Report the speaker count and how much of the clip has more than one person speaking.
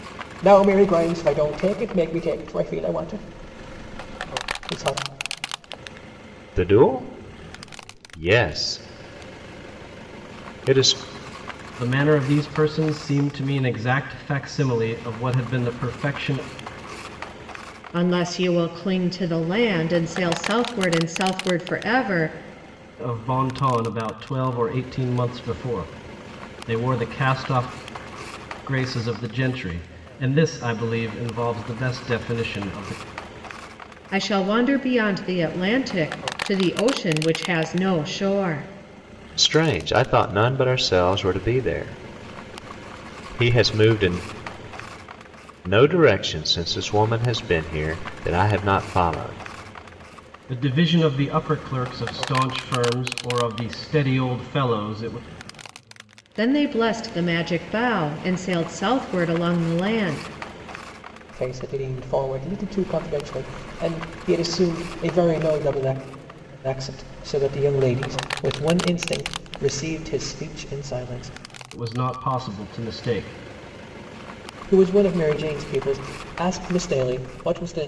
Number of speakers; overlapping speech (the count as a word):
four, no overlap